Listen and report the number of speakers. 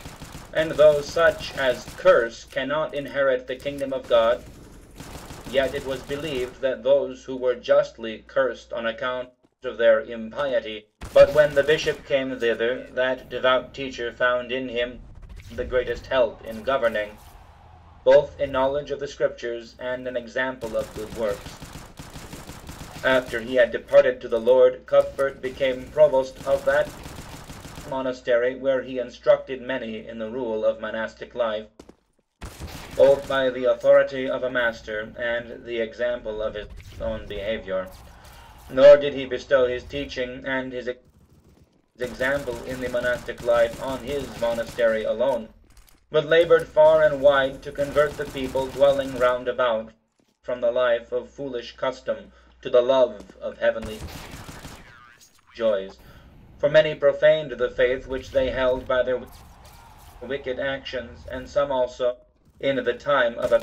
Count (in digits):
1